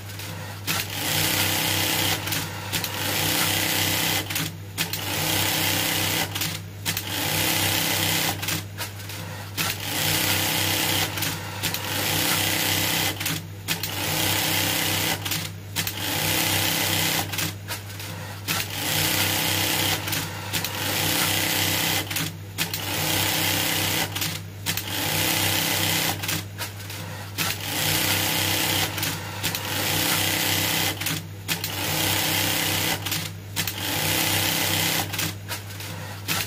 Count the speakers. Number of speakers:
zero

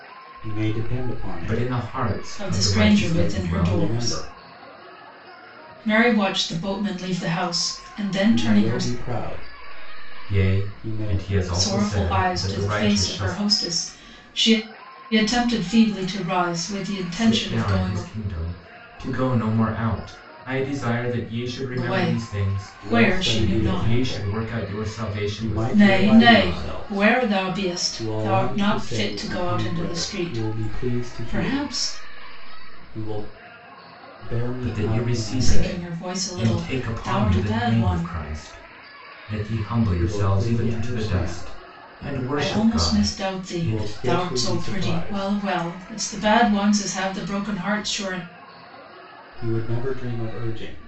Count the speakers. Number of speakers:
three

